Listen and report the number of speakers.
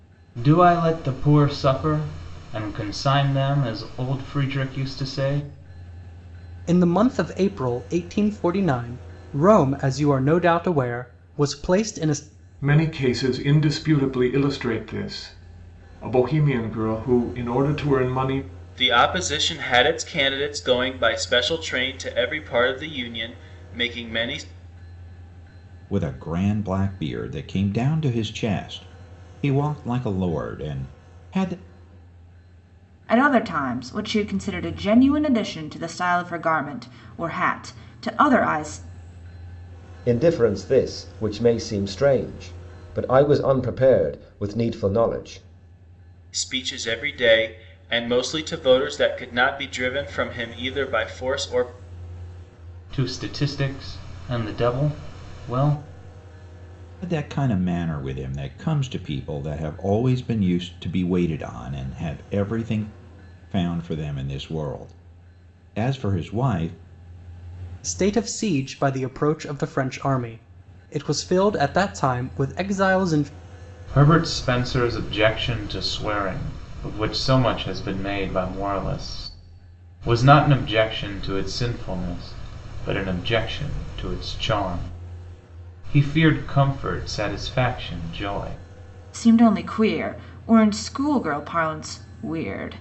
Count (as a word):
seven